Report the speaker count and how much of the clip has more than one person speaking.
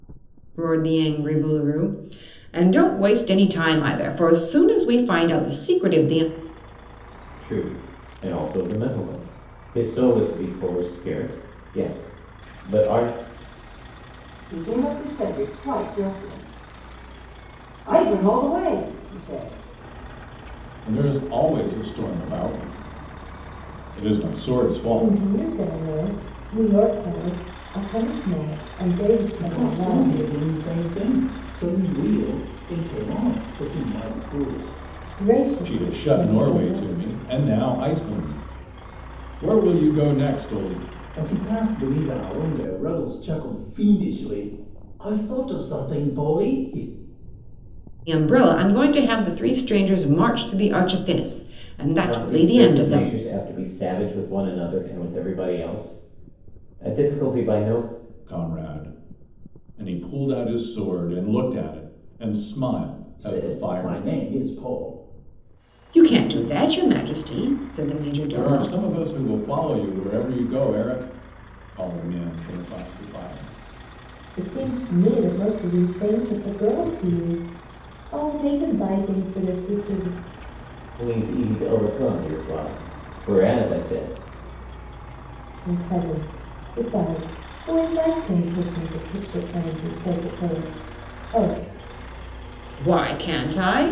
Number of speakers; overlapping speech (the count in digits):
6, about 5%